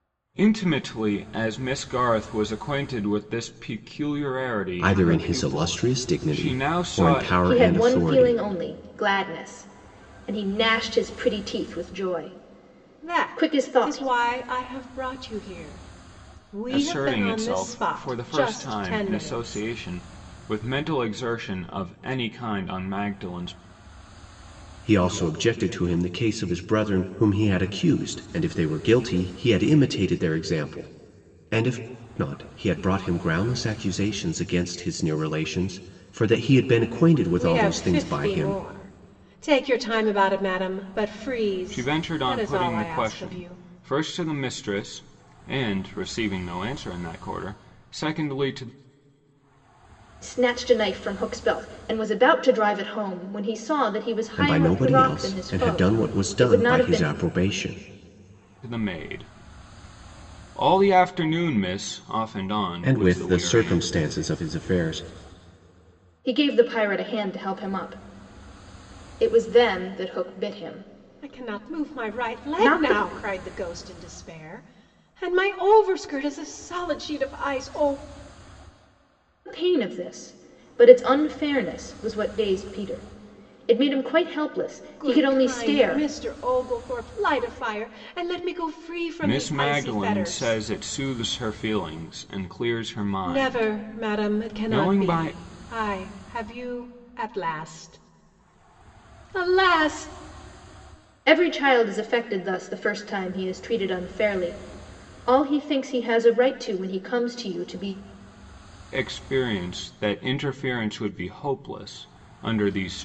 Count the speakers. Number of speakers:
four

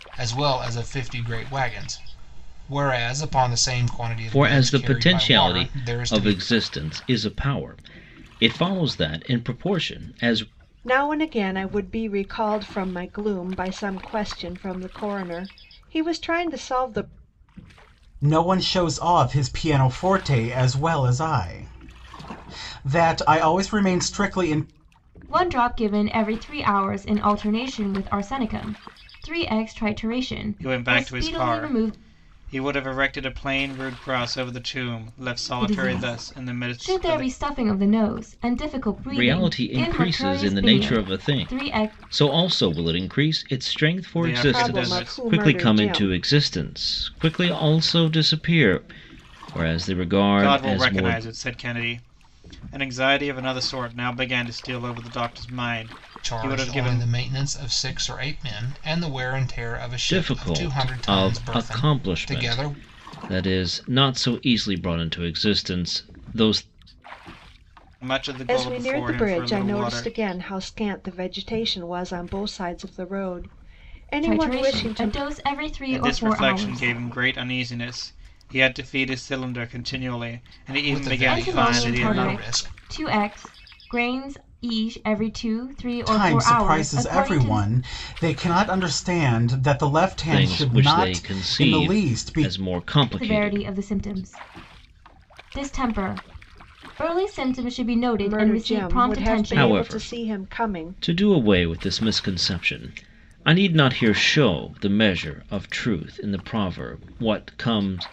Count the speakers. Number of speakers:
six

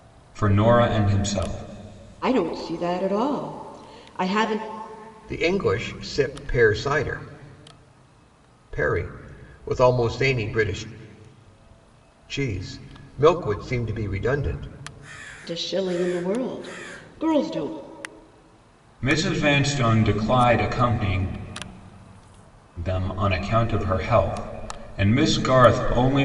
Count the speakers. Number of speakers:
three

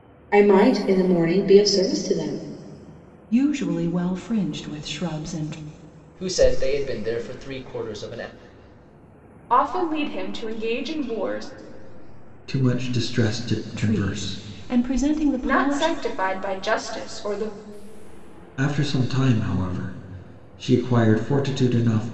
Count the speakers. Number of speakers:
five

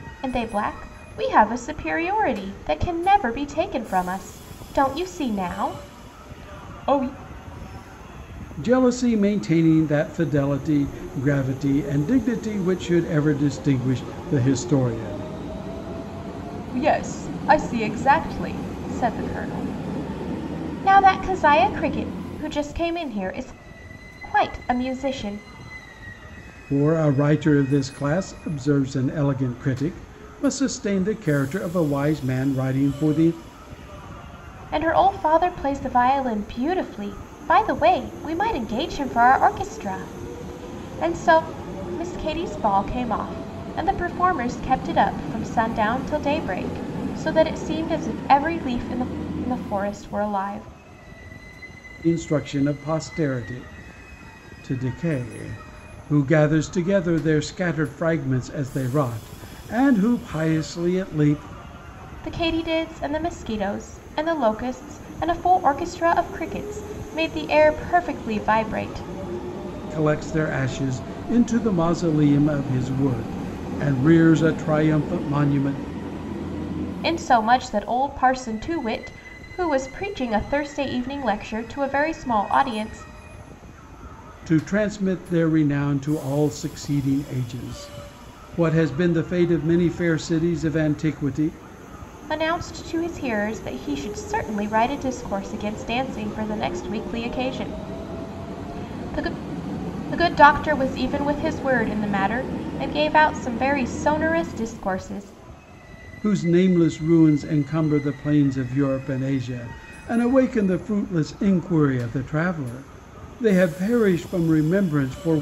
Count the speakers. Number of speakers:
two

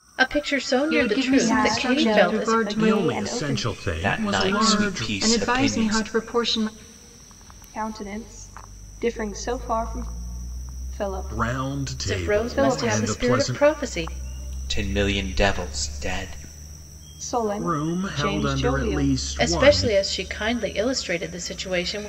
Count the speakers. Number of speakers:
five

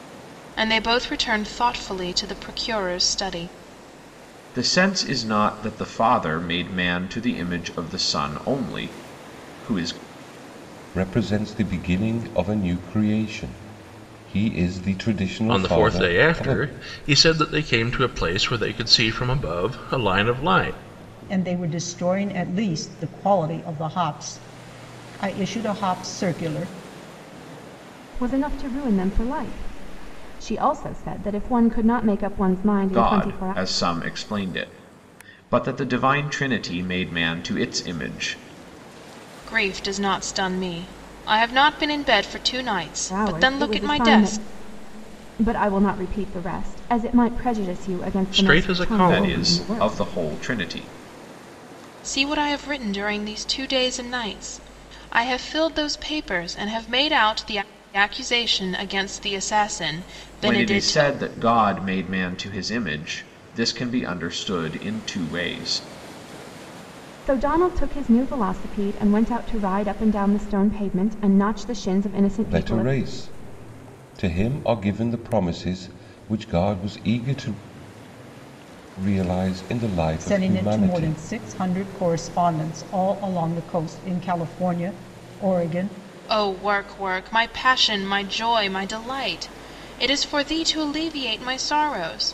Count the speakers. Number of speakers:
six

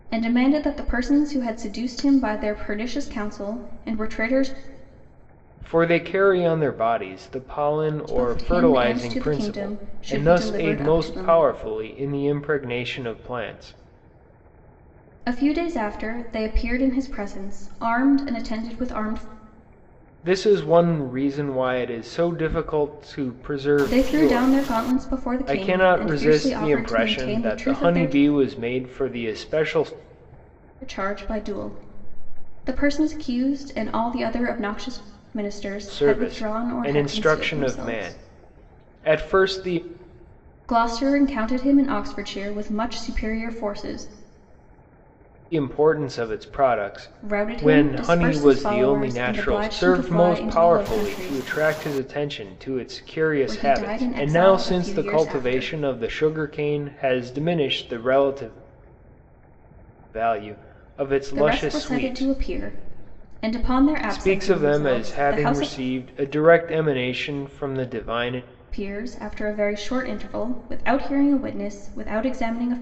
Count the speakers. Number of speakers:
two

